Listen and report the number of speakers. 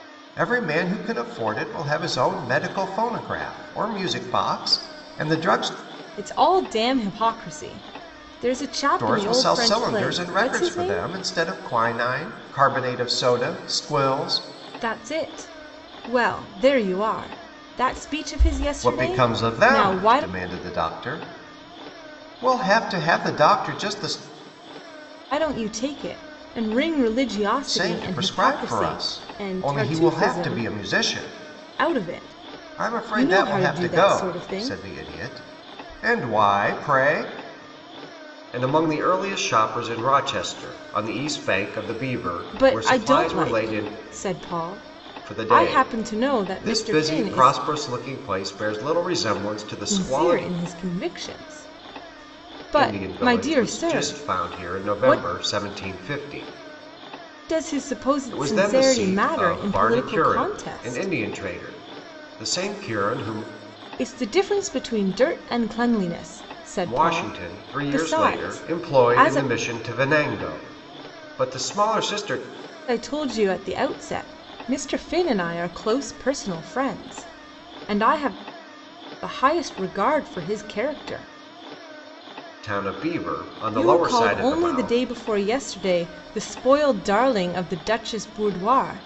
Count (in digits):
2